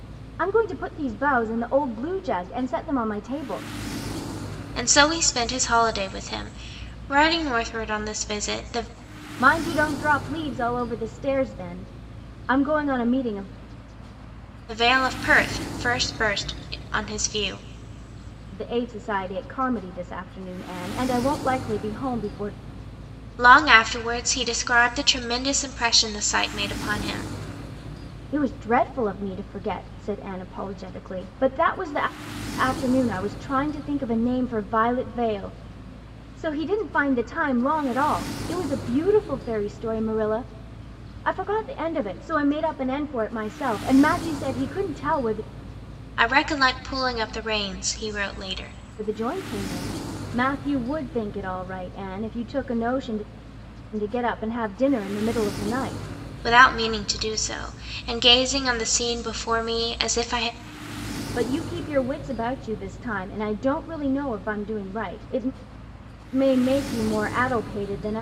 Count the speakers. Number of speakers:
2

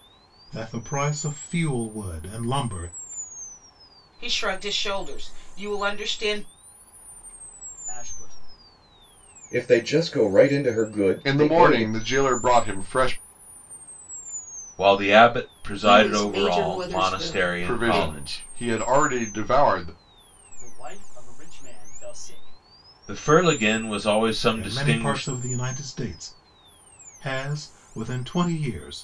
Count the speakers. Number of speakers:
7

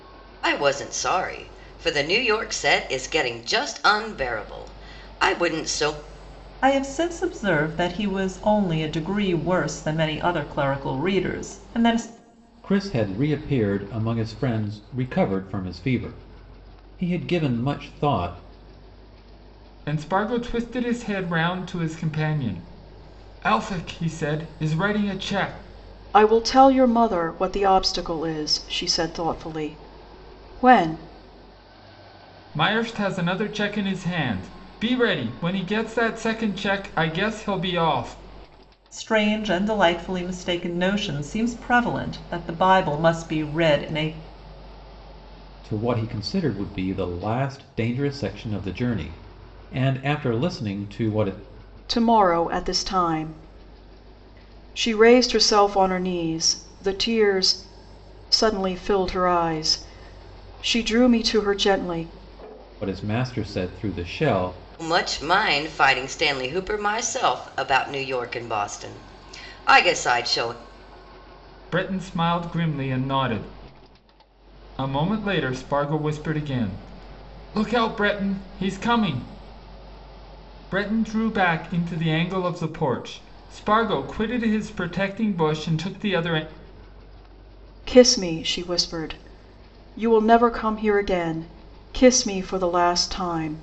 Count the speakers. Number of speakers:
5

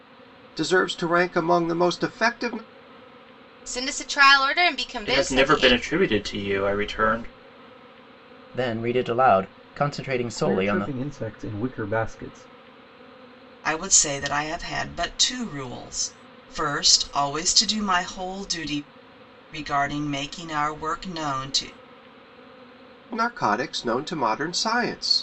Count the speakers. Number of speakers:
6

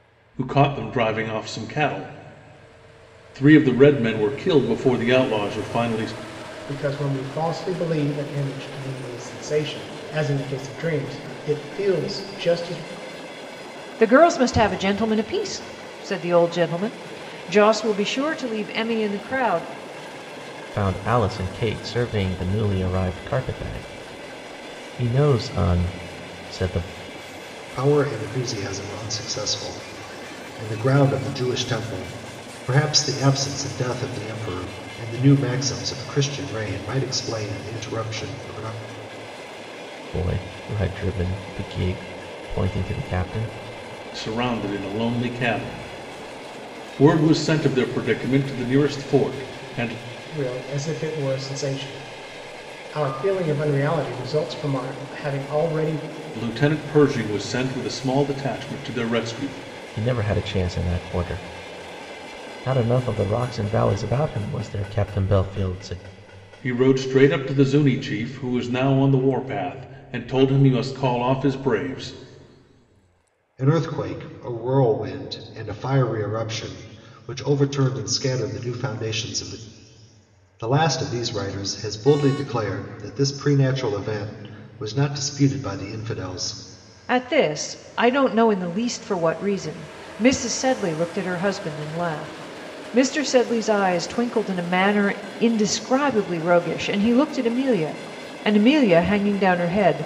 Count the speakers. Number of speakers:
5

